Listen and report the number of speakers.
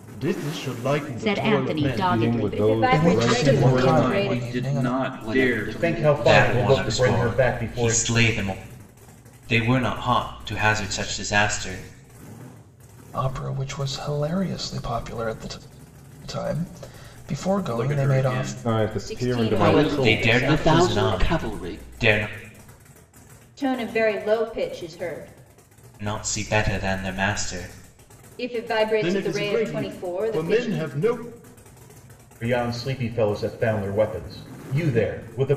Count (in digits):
9